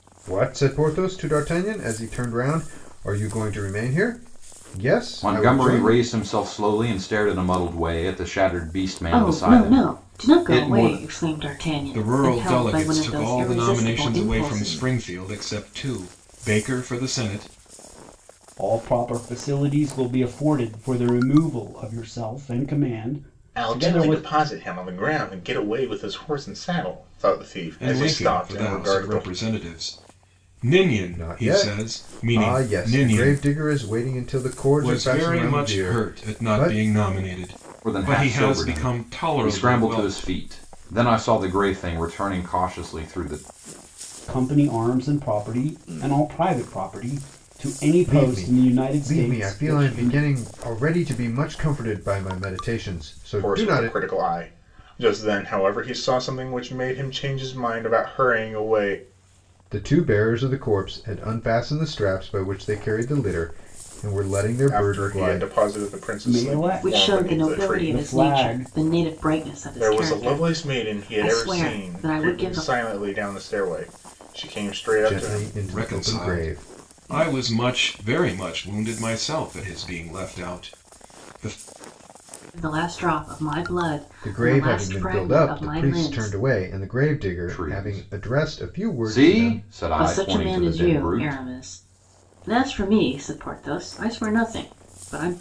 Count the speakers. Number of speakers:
6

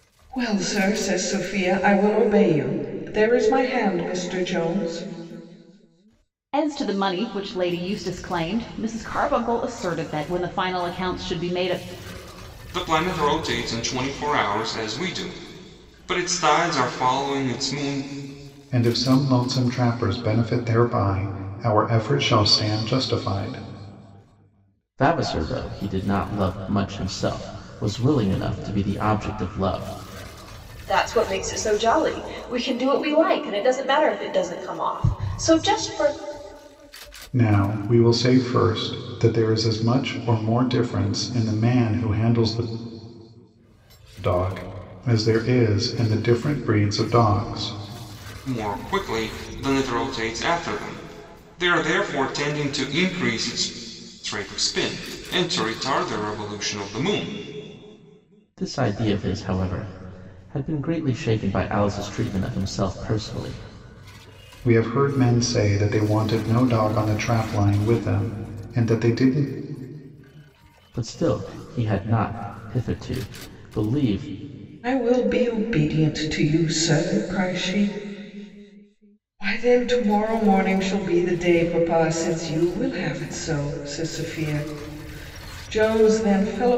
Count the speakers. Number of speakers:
6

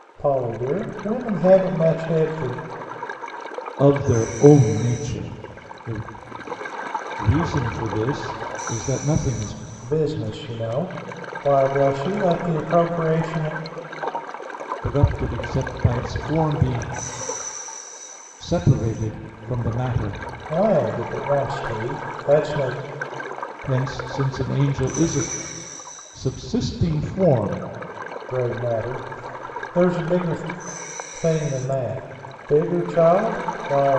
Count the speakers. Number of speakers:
2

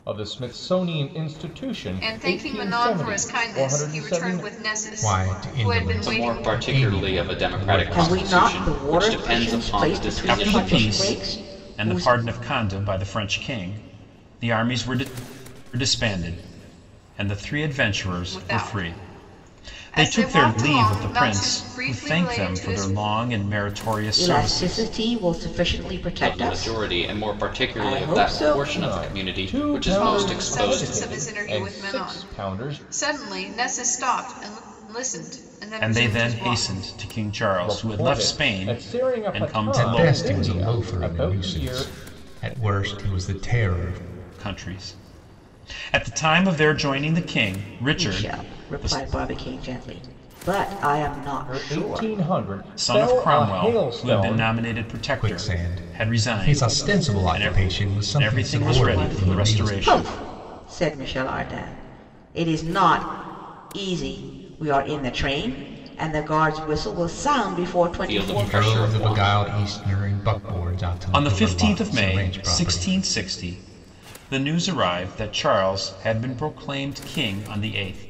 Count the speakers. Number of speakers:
6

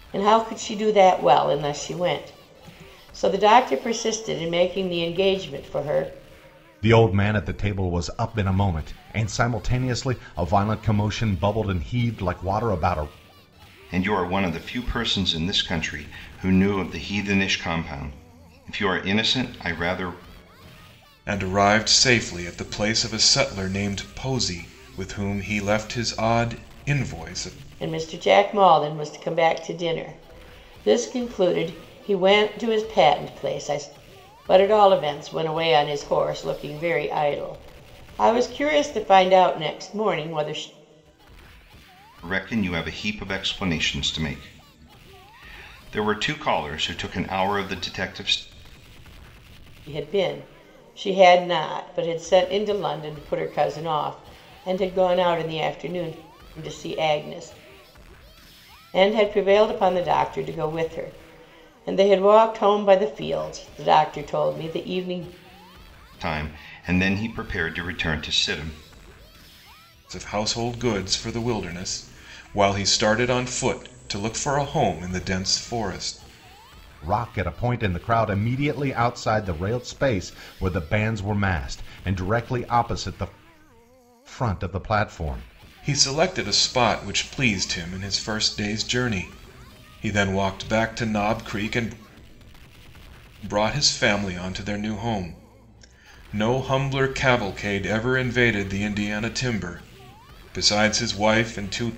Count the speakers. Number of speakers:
4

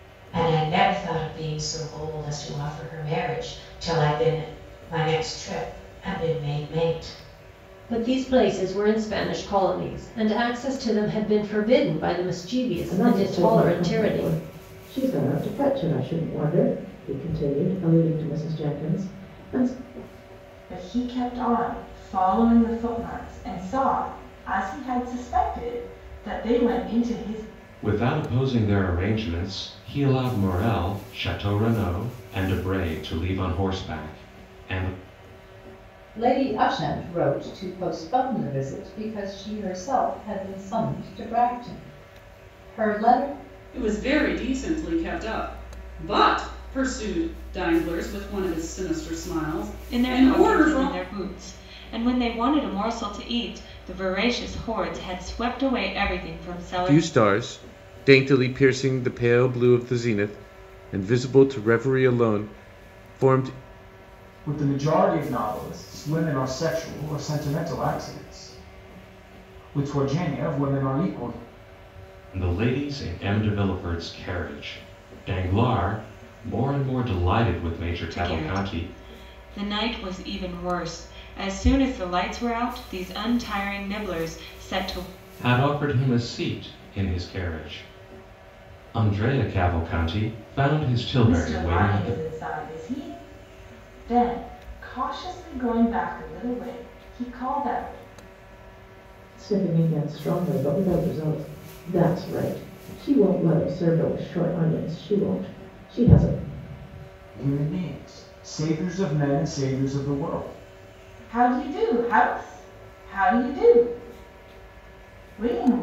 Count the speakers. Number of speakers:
10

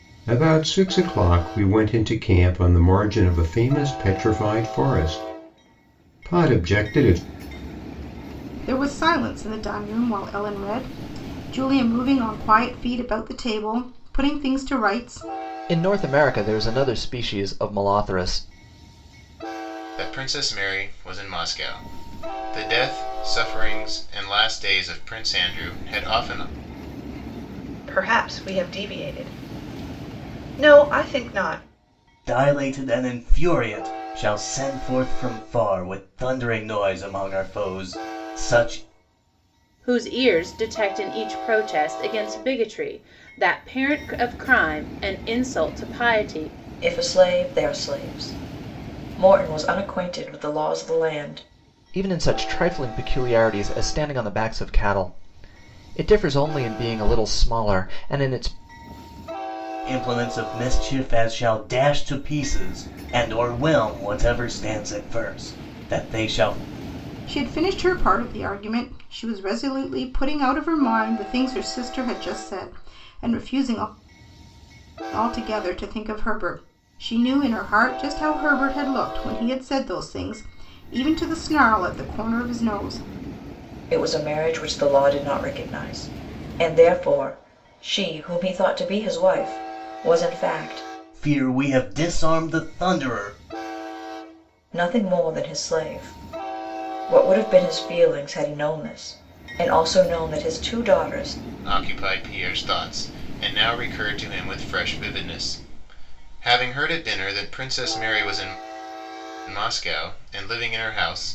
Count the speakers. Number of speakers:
8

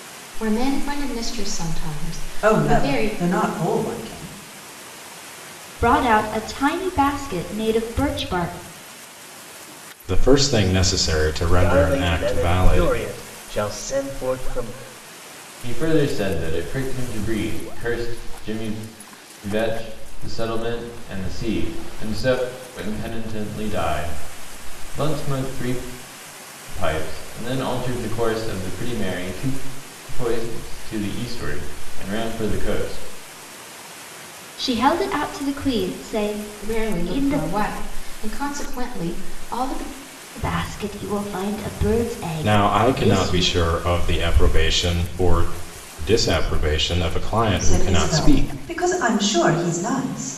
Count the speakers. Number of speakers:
6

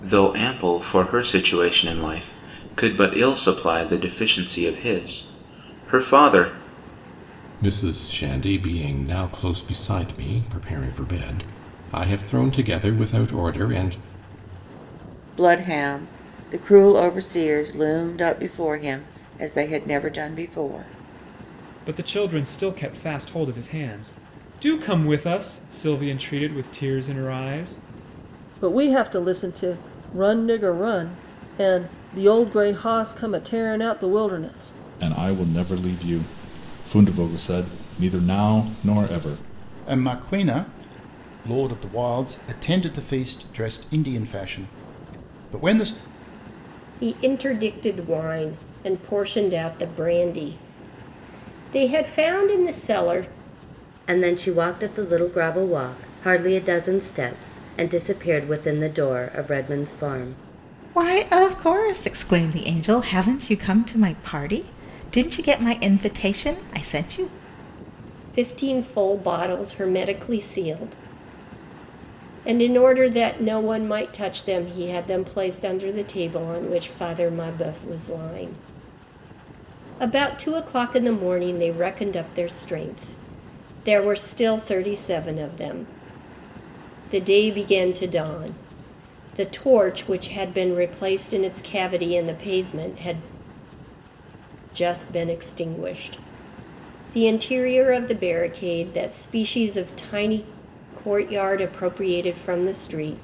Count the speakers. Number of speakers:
10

